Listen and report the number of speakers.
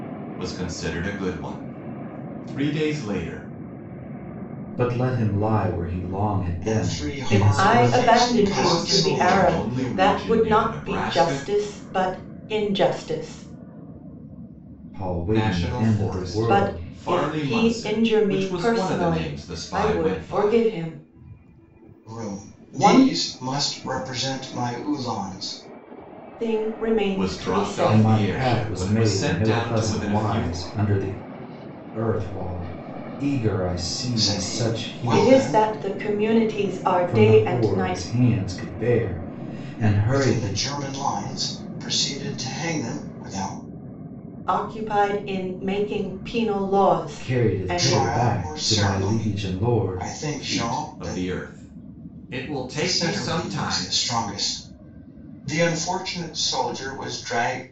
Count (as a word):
four